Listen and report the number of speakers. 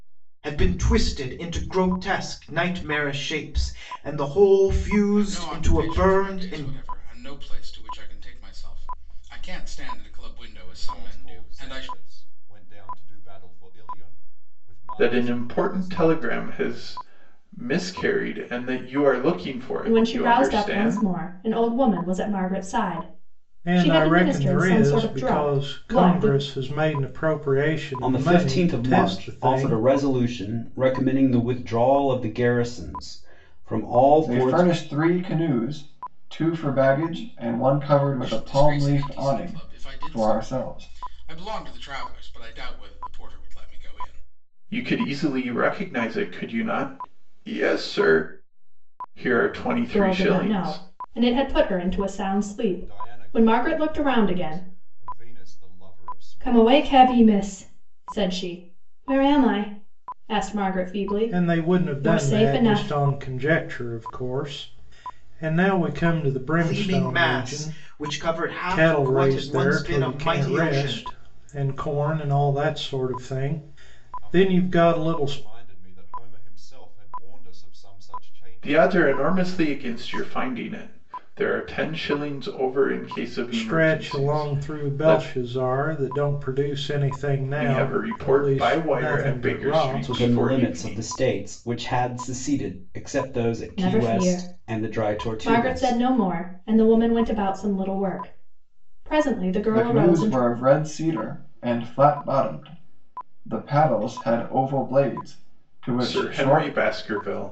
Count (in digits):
8